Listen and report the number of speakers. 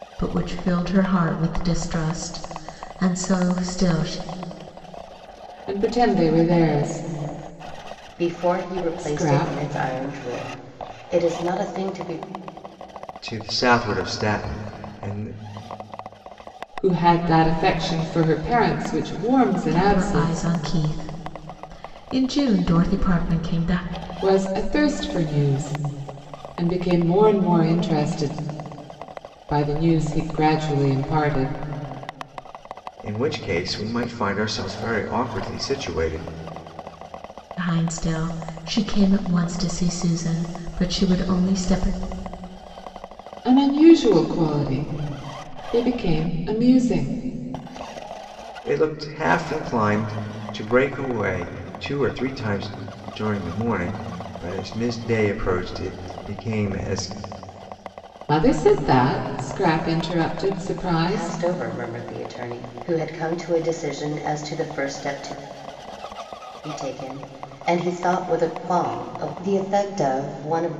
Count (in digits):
4